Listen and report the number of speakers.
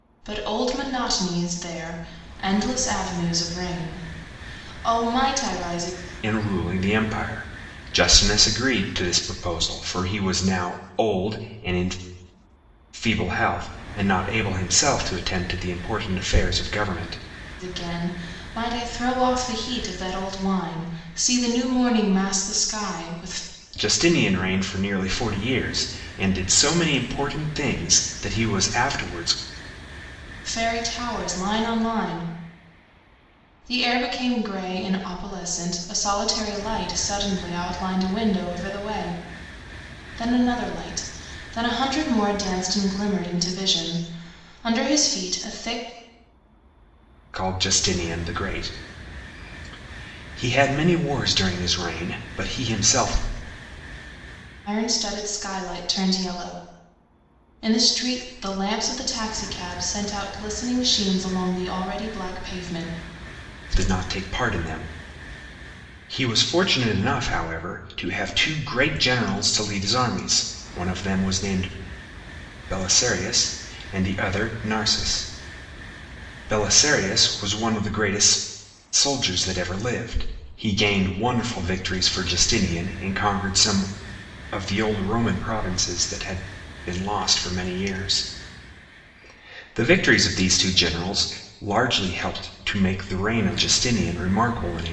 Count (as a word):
two